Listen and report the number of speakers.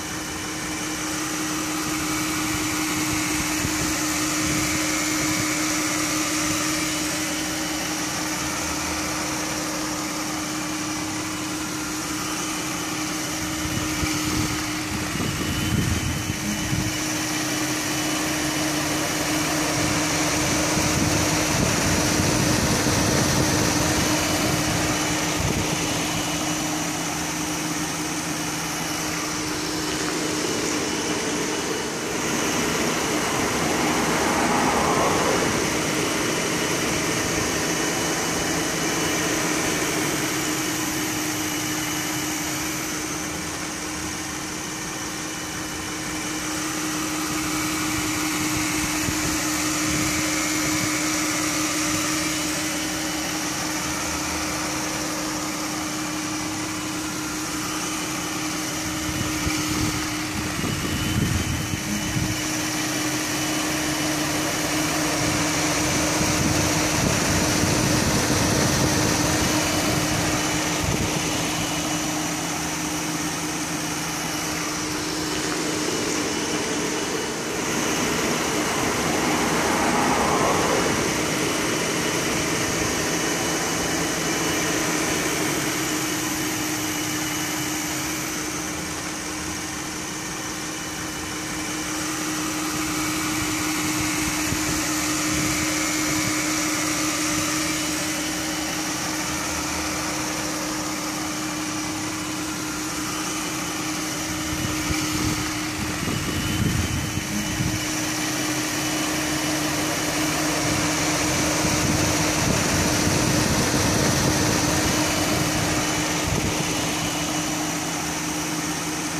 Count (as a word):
zero